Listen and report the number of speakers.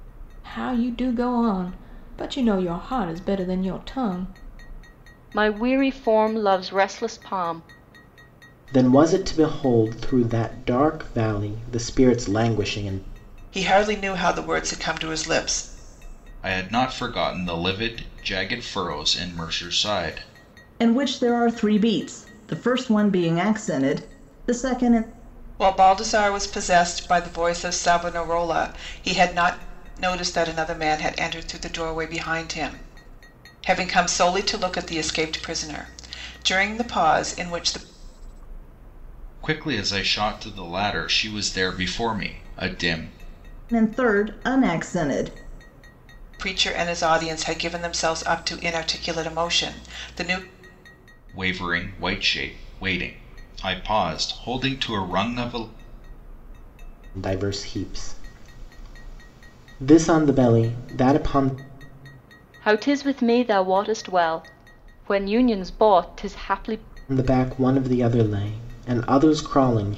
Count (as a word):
six